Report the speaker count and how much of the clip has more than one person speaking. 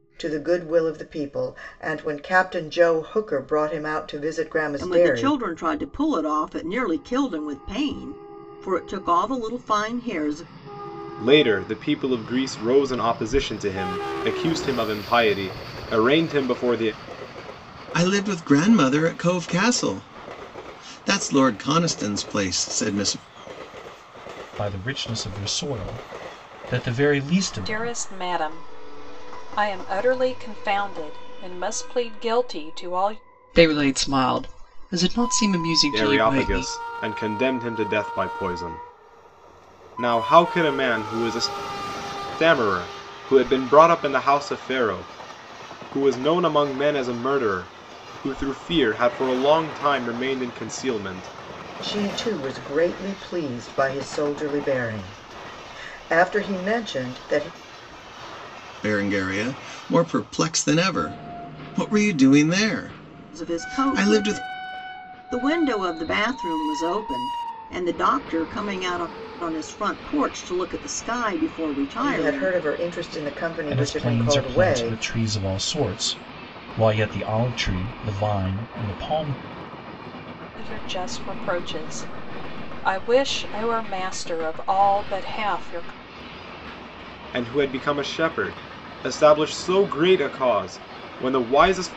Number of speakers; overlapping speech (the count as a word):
seven, about 5%